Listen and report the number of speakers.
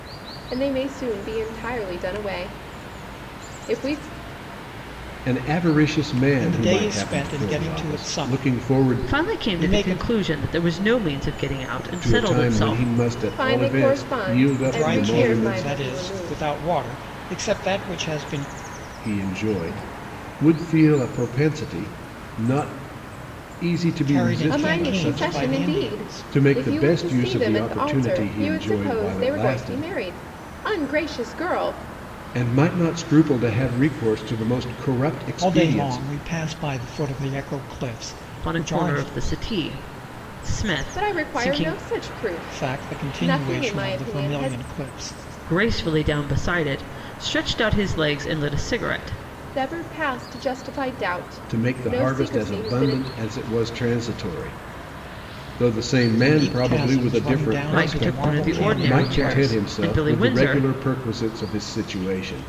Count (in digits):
4